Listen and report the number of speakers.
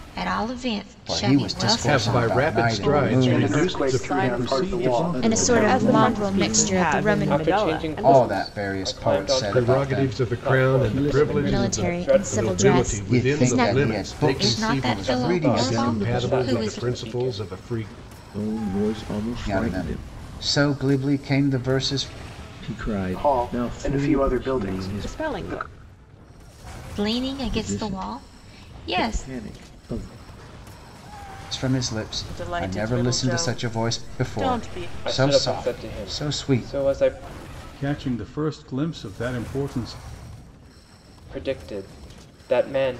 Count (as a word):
ten